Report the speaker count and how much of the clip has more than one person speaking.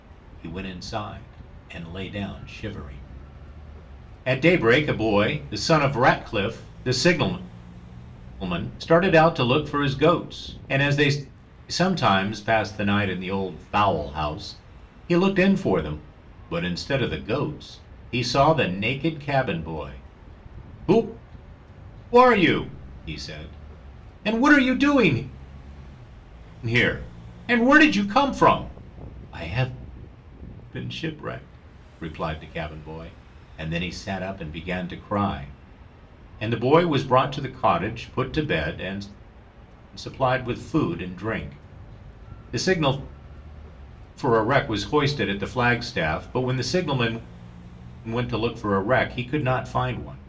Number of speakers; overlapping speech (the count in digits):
1, no overlap